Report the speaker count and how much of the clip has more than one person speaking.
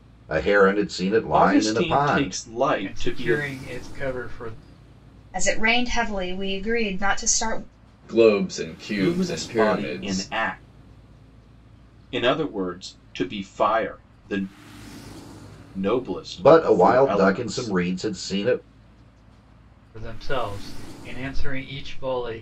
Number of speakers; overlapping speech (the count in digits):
5, about 20%